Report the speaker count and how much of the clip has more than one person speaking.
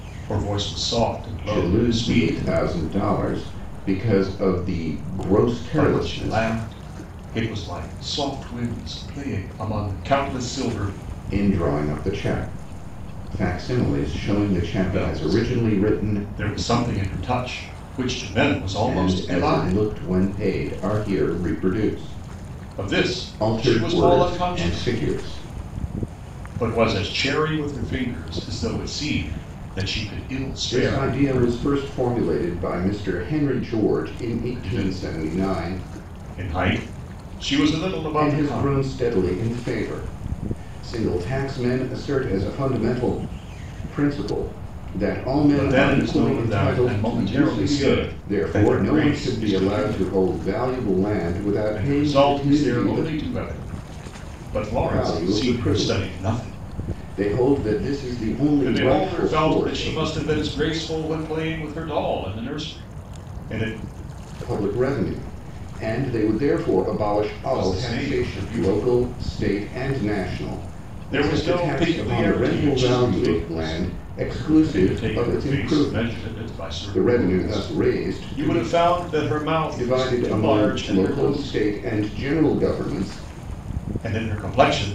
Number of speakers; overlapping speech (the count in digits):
2, about 34%